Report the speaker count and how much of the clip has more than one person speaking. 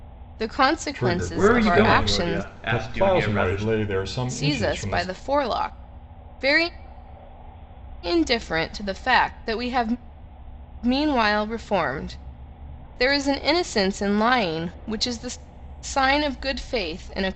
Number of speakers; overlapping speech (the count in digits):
3, about 21%